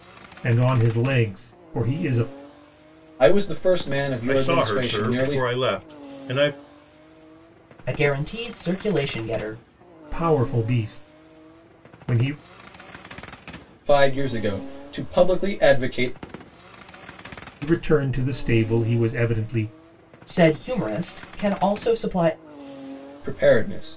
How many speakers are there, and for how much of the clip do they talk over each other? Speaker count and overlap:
4, about 5%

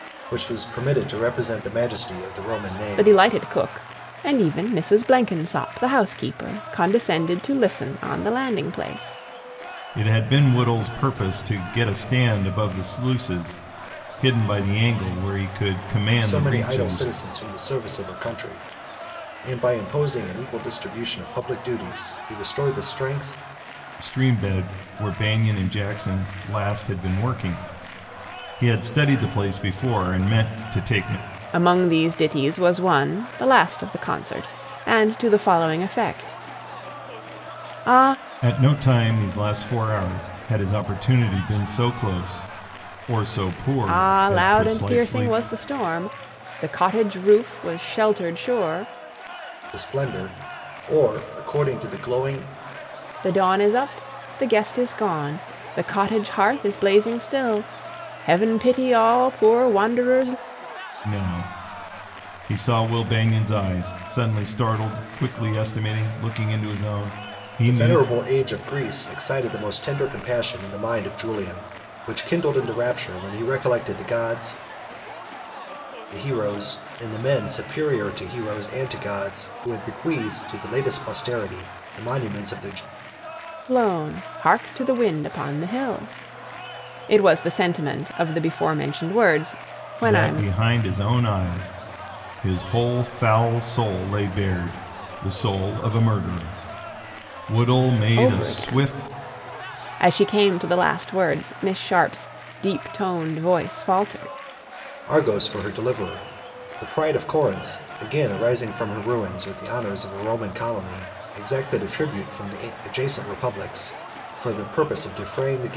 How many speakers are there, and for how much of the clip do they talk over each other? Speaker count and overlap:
3, about 4%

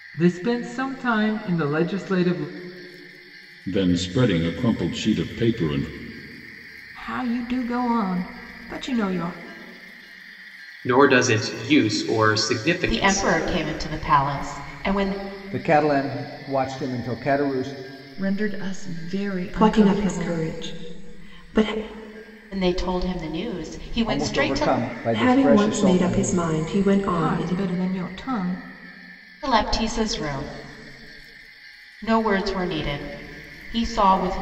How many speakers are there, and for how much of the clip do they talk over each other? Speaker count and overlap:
8, about 11%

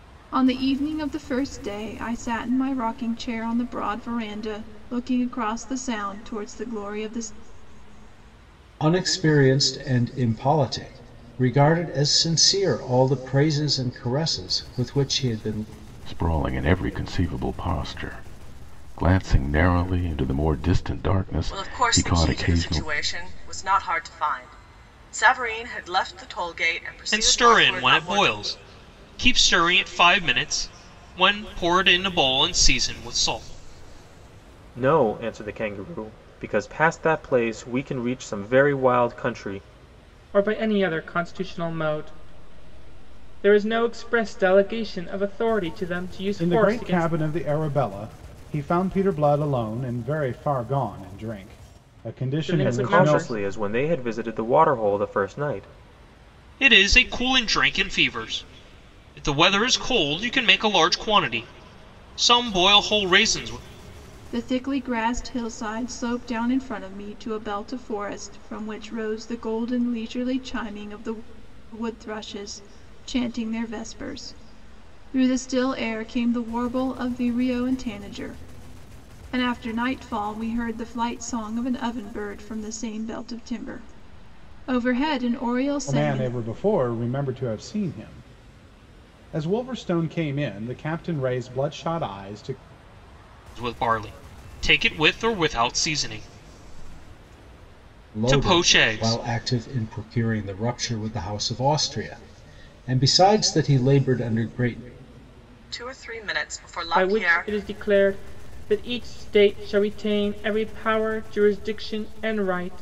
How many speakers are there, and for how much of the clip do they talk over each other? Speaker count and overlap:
8, about 6%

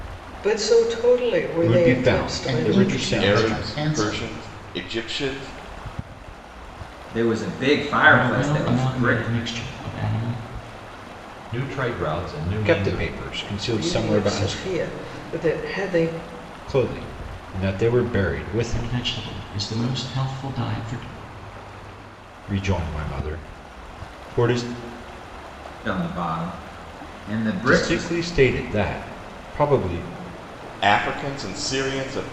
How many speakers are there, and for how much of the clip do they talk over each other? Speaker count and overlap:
7, about 19%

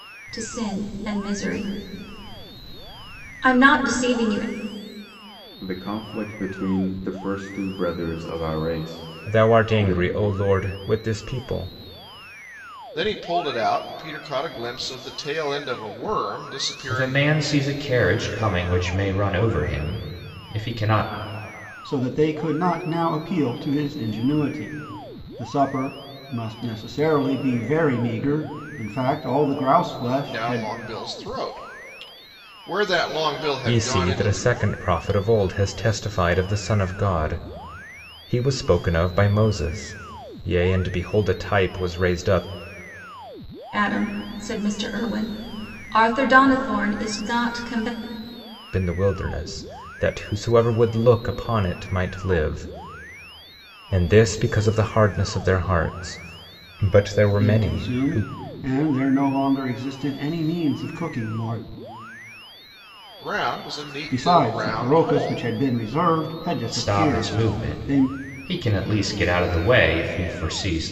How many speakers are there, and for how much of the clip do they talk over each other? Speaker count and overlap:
6, about 9%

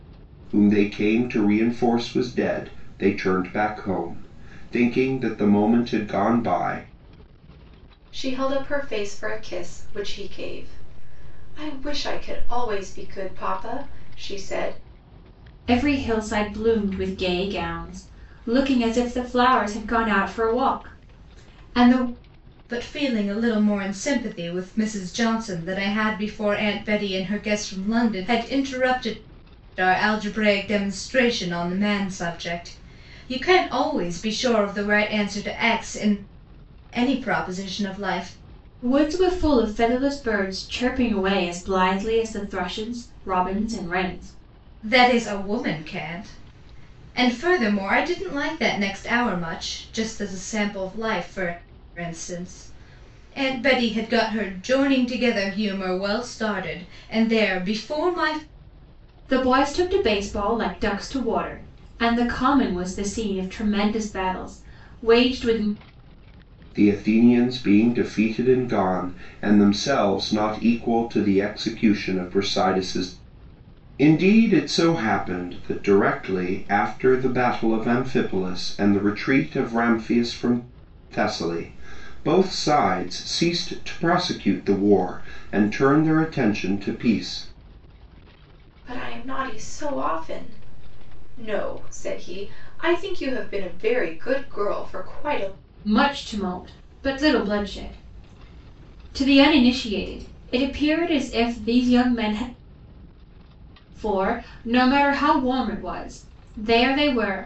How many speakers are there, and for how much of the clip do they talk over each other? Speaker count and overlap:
4, no overlap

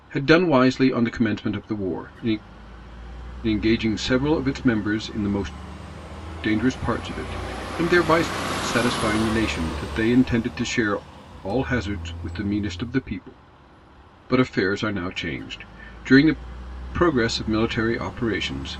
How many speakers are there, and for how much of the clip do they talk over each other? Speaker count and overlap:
1, no overlap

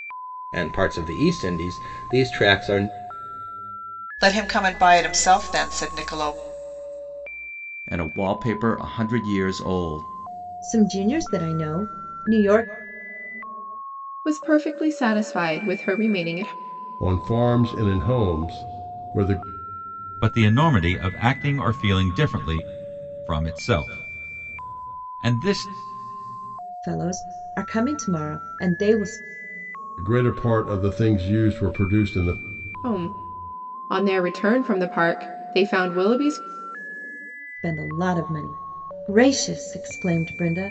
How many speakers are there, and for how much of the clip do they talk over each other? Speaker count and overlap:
7, no overlap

